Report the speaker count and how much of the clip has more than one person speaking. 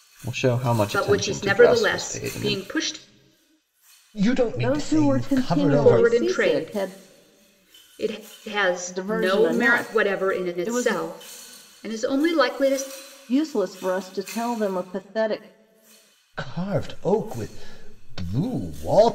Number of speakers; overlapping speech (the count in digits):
4, about 33%